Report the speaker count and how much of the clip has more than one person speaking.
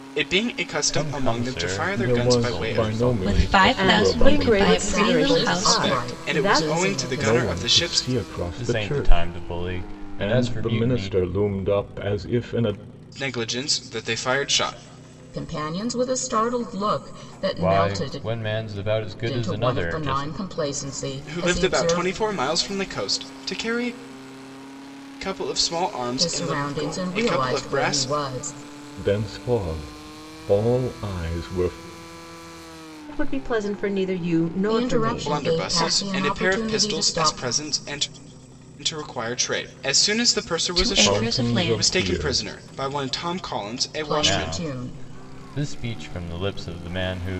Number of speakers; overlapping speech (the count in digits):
6, about 41%